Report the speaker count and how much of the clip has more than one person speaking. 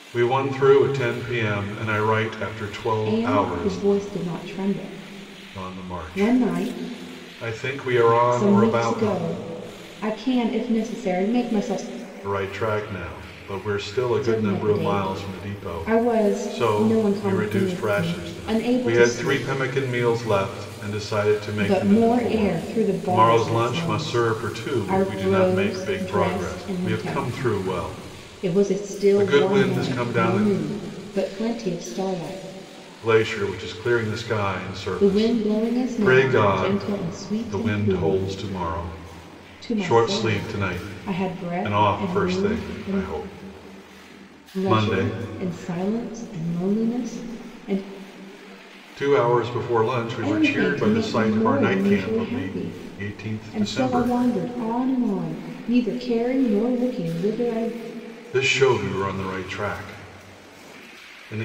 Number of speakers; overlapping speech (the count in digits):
2, about 42%